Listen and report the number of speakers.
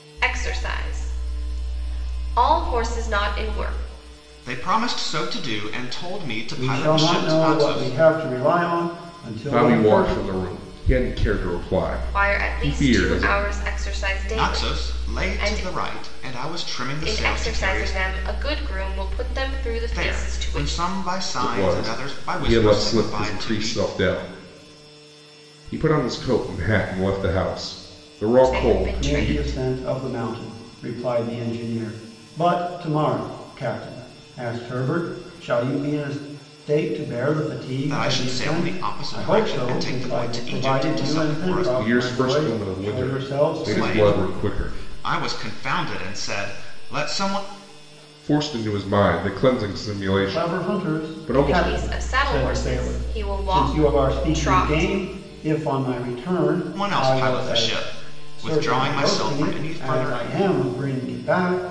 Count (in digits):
4